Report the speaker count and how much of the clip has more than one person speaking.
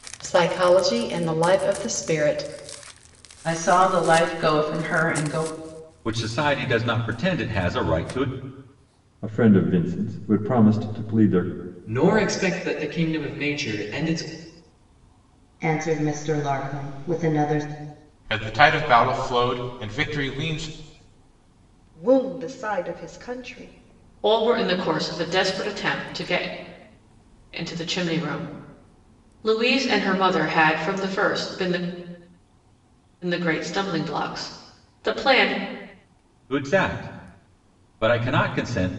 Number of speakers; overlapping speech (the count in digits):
9, no overlap